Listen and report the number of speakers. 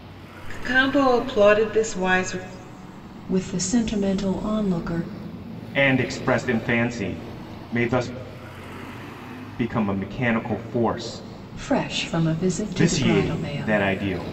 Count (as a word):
three